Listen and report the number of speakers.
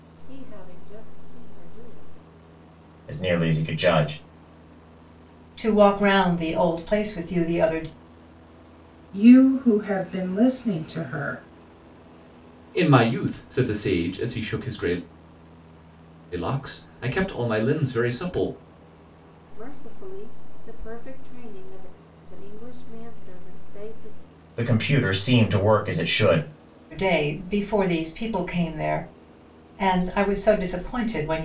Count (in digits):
5